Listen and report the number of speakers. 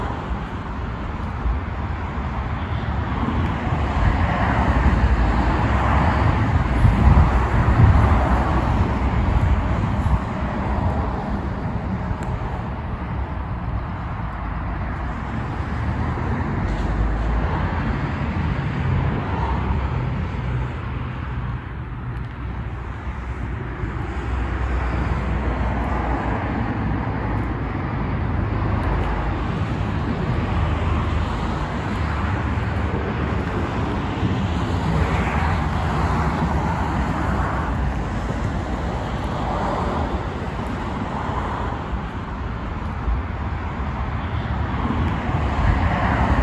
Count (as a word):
zero